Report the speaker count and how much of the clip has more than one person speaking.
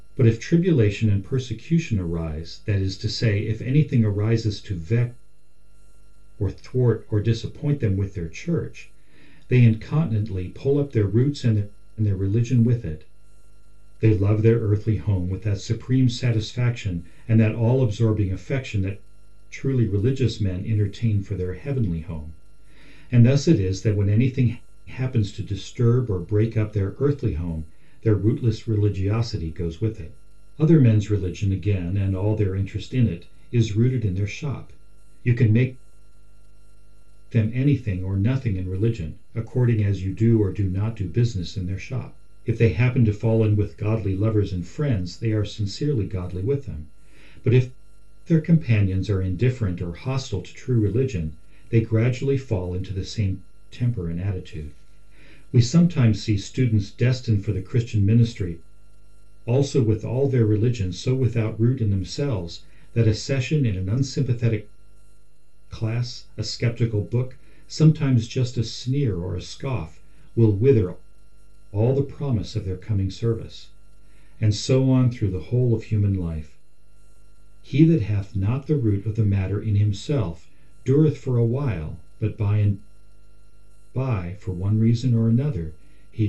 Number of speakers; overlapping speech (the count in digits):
1, no overlap